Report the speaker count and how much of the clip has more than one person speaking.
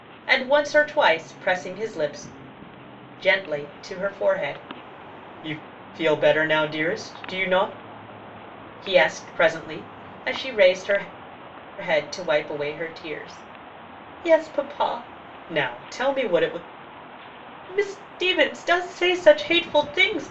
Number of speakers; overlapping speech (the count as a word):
one, no overlap